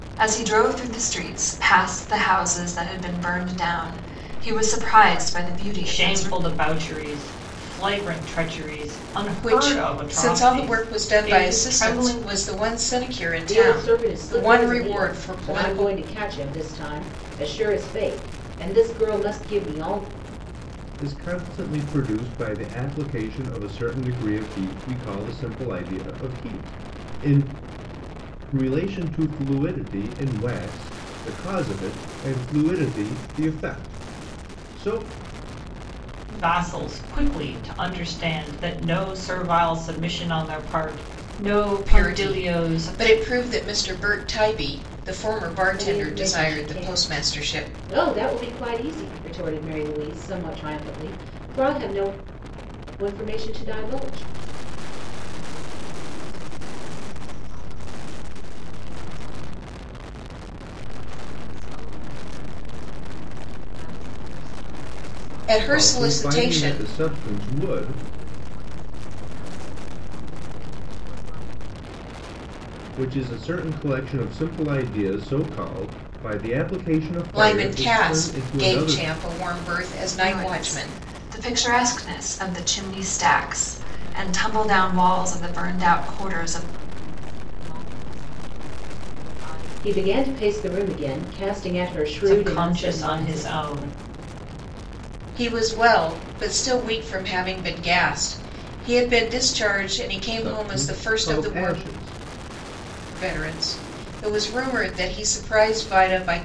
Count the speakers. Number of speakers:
six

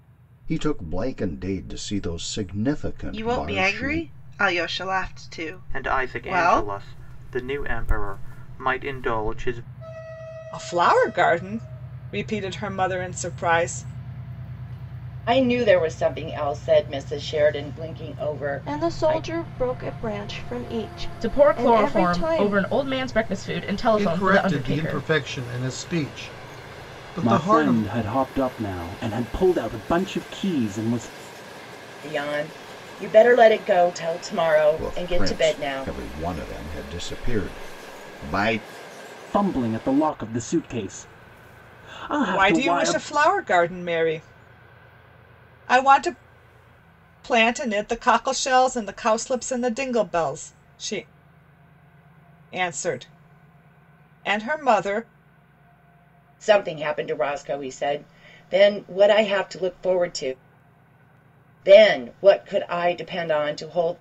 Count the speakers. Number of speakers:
nine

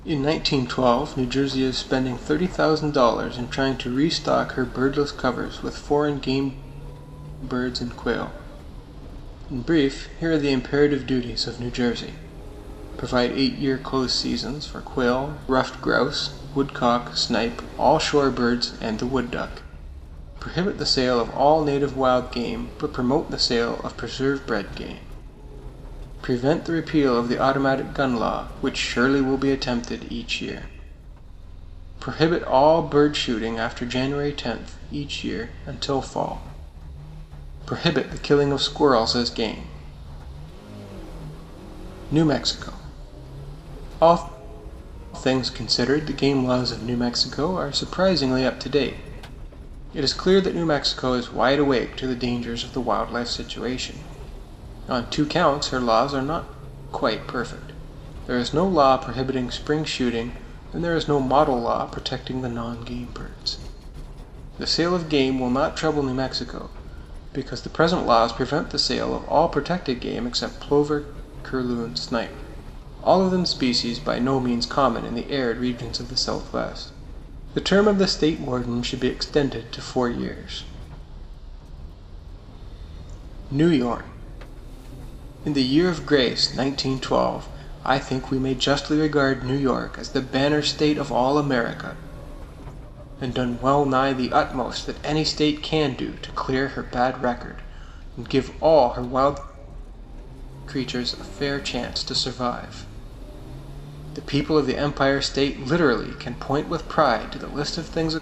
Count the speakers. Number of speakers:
one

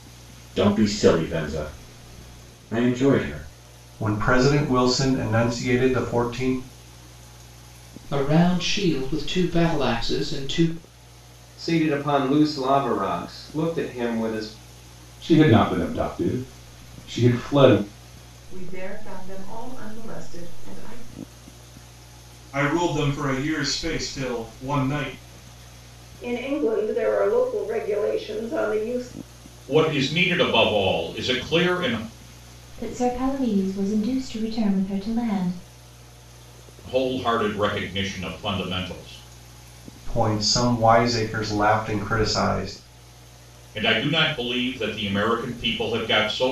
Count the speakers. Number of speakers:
ten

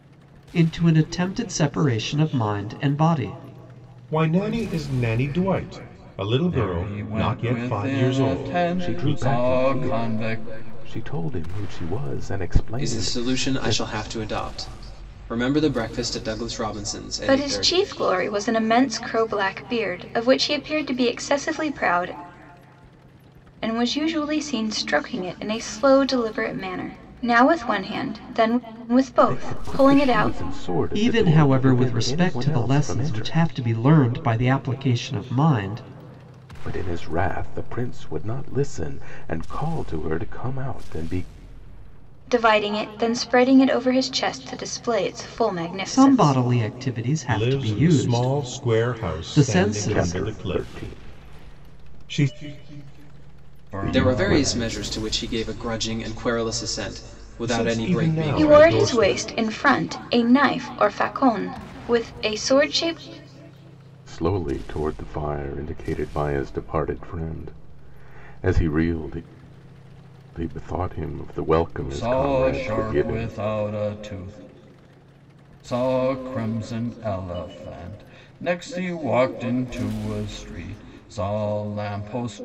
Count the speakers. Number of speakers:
six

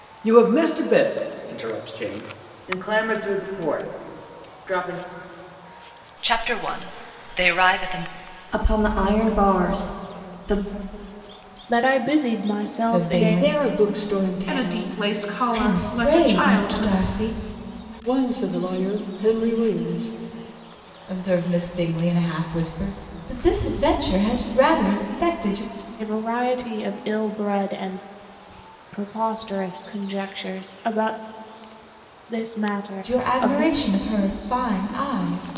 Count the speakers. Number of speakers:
eight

